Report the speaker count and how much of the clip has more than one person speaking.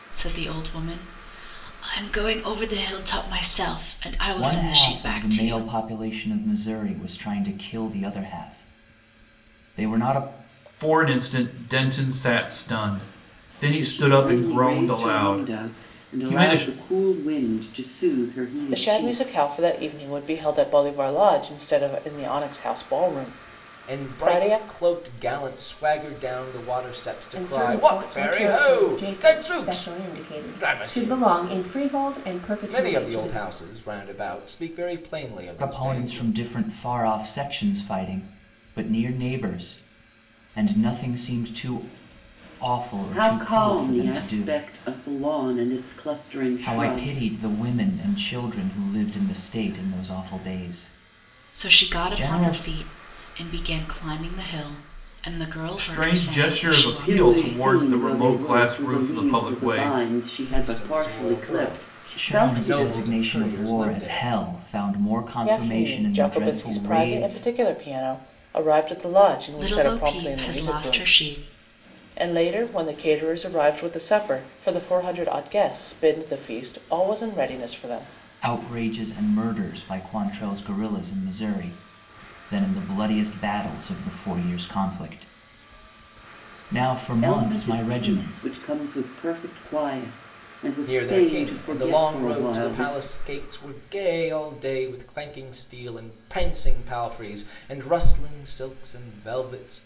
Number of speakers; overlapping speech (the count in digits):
7, about 30%